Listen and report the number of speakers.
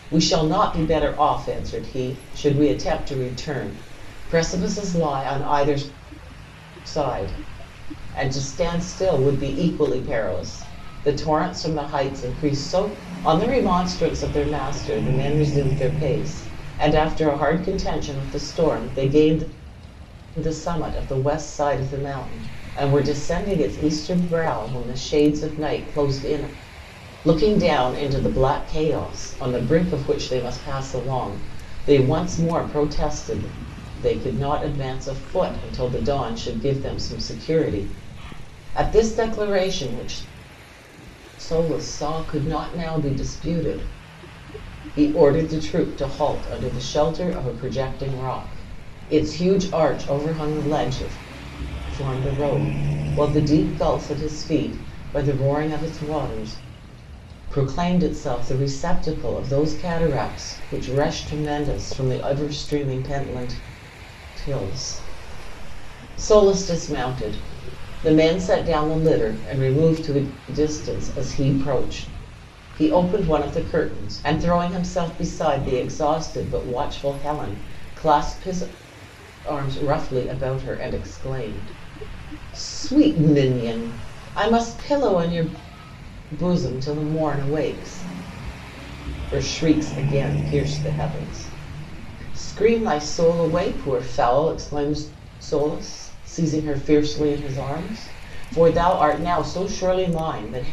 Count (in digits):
1